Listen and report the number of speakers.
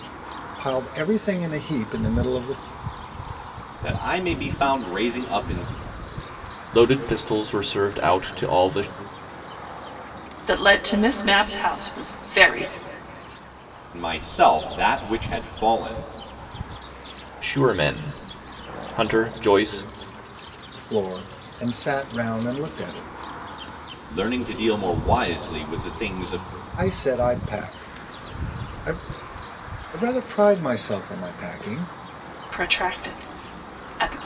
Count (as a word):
four